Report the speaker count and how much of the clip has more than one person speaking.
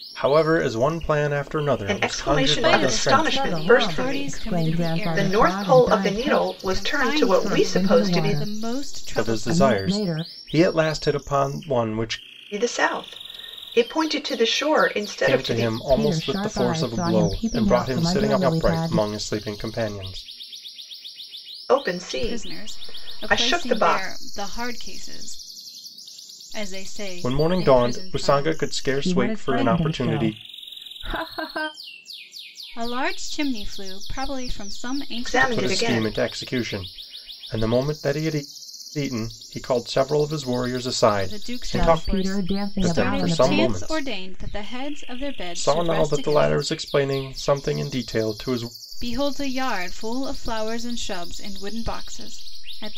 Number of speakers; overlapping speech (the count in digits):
4, about 42%